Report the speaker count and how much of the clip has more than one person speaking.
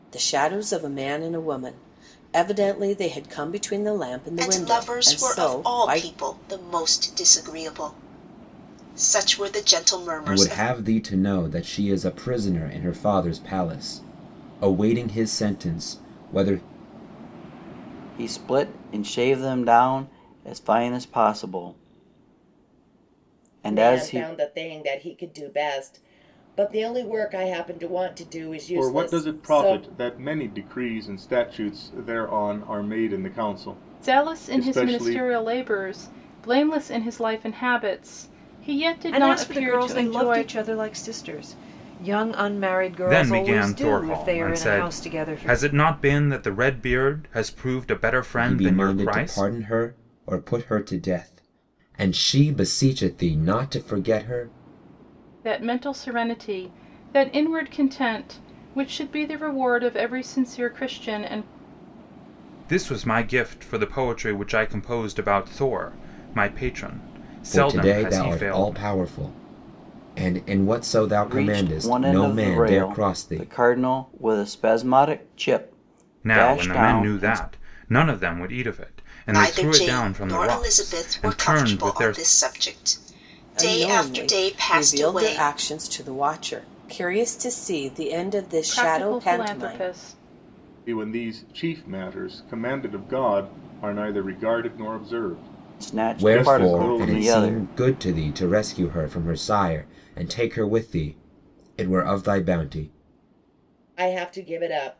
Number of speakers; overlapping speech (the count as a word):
nine, about 22%